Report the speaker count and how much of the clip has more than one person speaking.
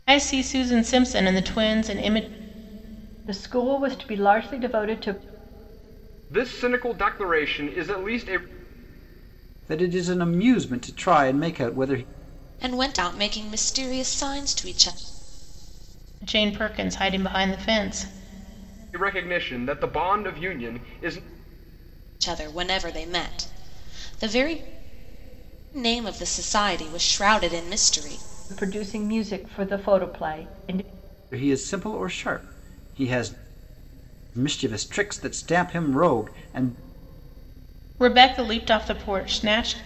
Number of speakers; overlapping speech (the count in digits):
5, no overlap